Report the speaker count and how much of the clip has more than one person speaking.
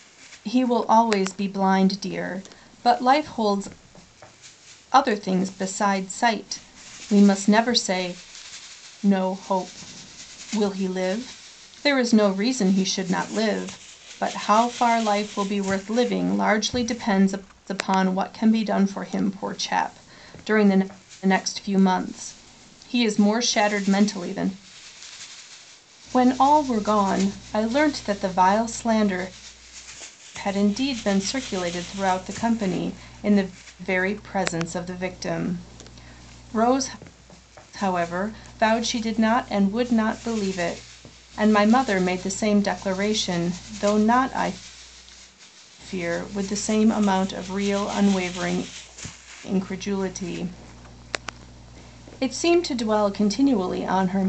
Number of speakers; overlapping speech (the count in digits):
1, no overlap